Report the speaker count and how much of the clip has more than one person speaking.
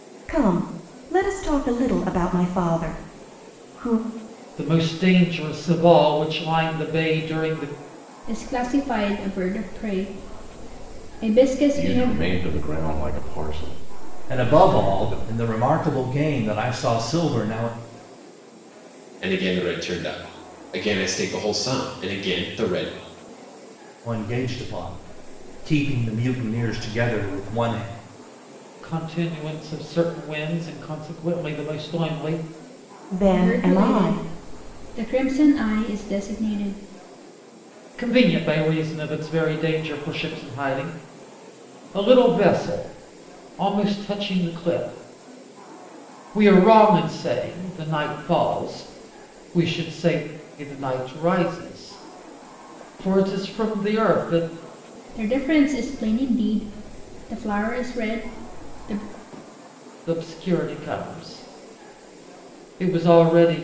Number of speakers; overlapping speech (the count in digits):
6, about 4%